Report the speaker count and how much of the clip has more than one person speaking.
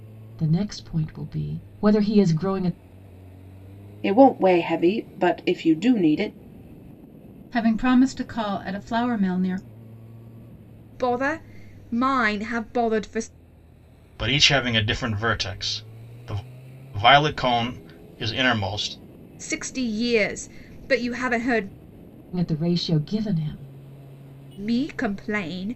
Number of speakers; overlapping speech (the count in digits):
5, no overlap